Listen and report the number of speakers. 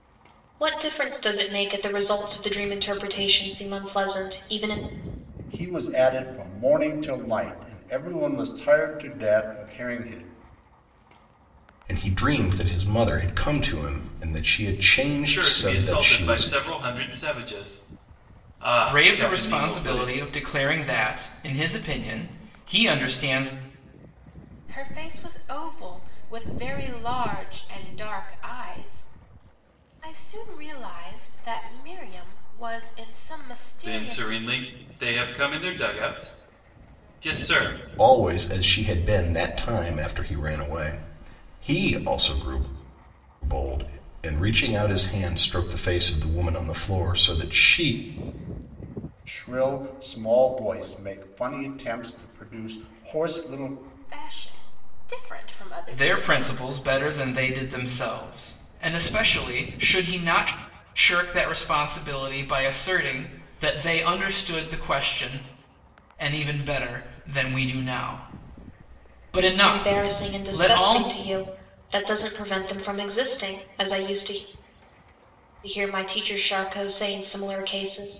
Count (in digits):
6